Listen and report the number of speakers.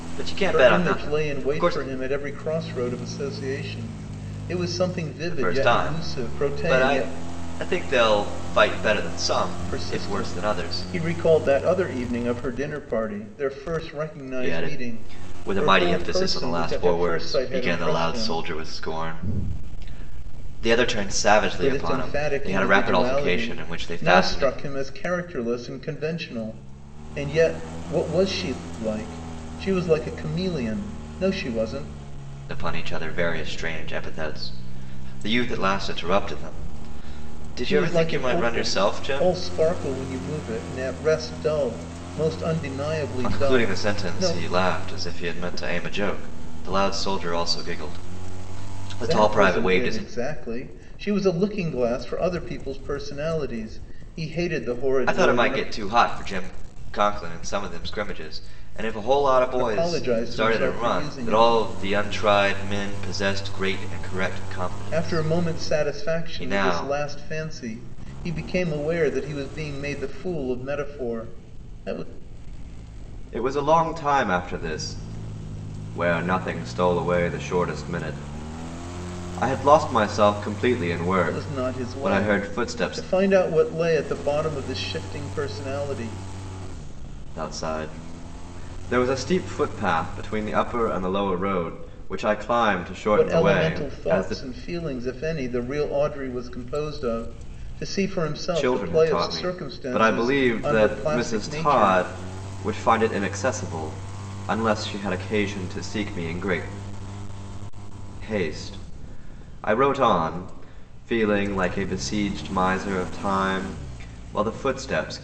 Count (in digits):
2